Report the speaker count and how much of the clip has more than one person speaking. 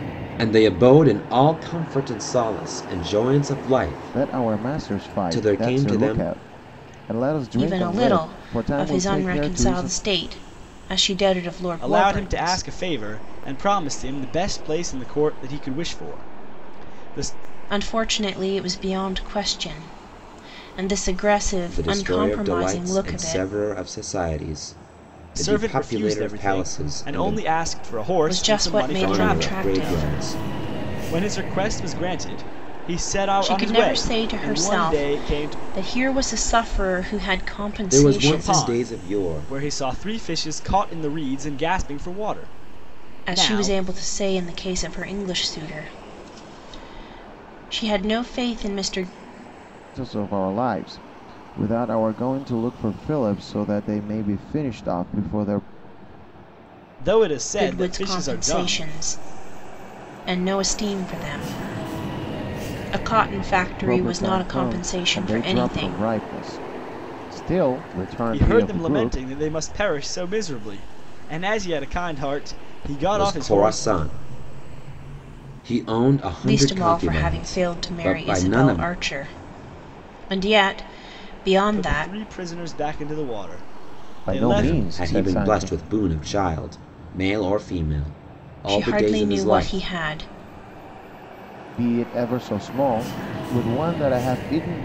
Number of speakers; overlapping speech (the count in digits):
4, about 29%